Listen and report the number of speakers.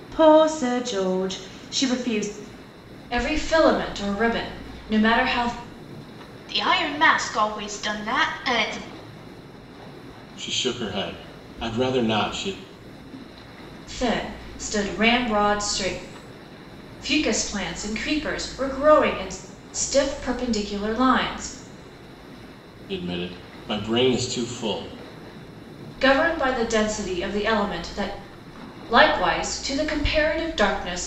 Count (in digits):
4